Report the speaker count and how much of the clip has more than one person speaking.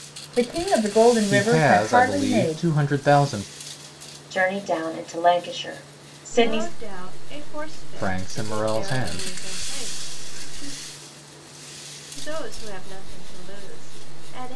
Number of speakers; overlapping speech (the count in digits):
4, about 23%